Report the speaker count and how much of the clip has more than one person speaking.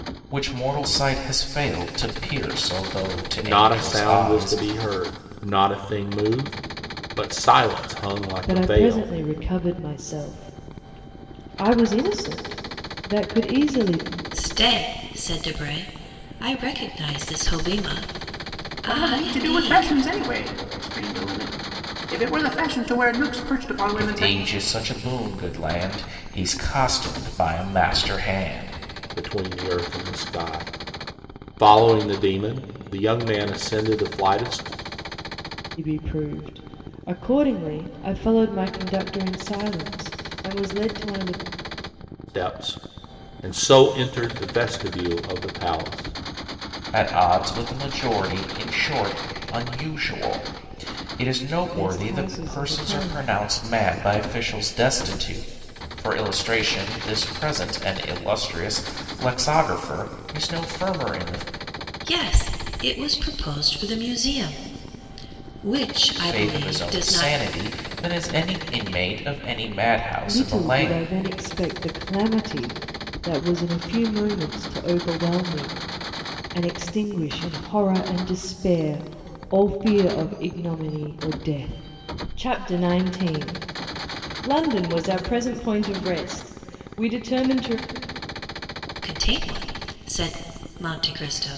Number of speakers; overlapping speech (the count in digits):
5, about 8%